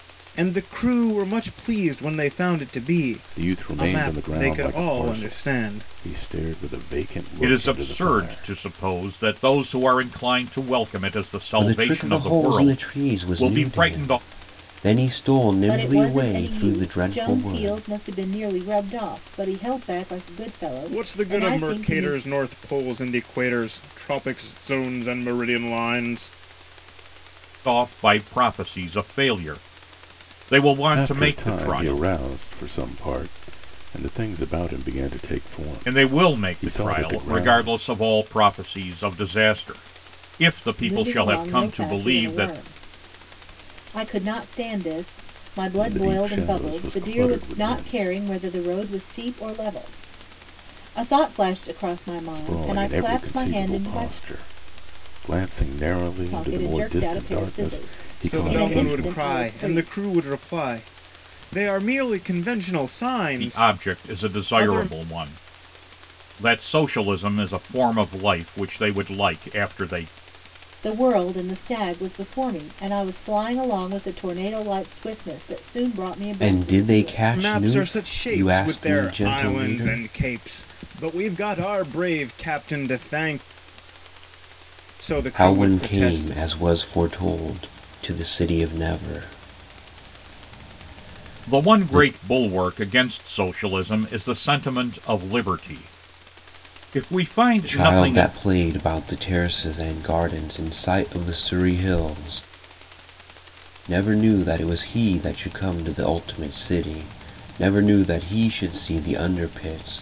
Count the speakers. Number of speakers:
5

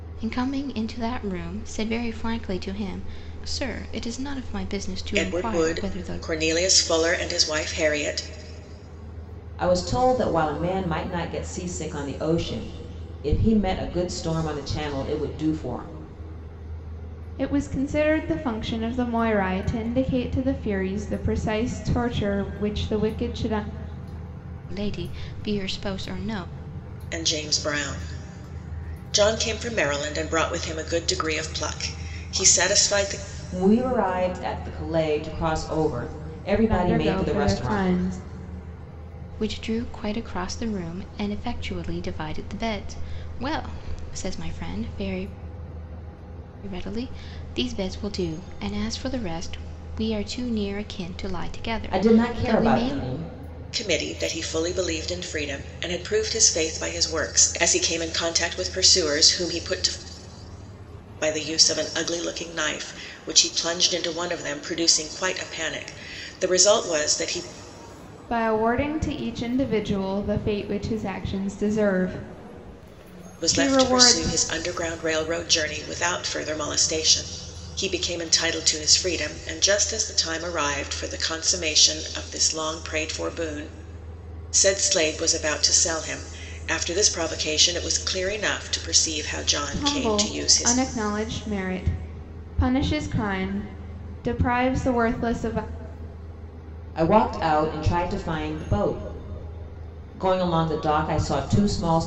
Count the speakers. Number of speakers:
4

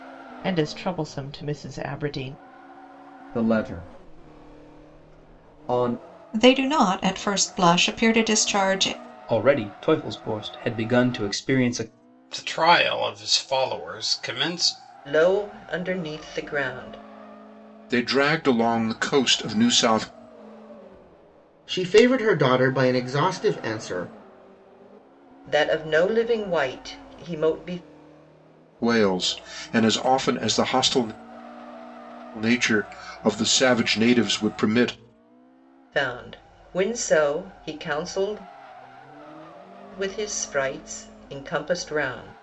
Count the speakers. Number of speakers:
8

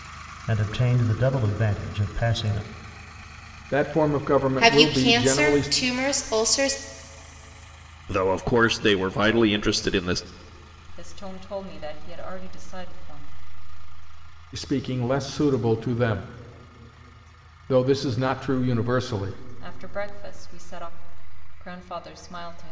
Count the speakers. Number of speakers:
5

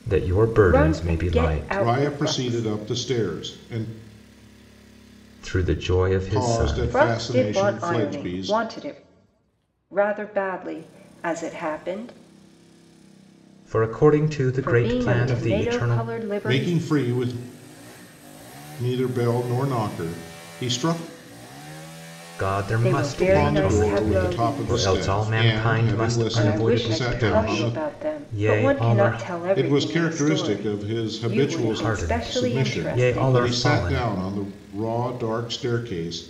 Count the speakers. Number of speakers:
3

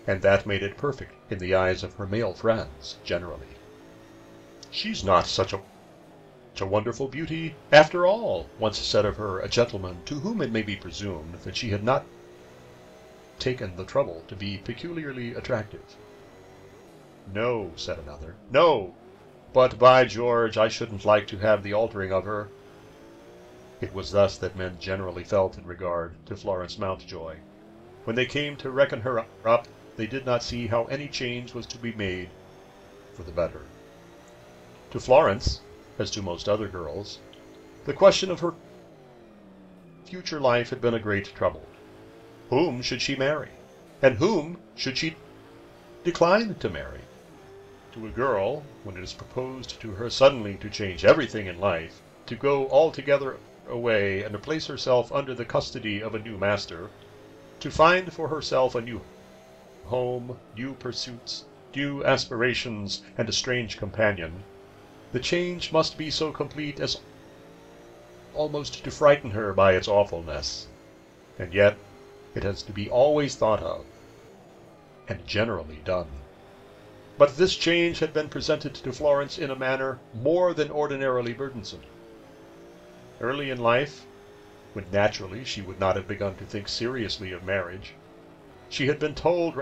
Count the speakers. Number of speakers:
1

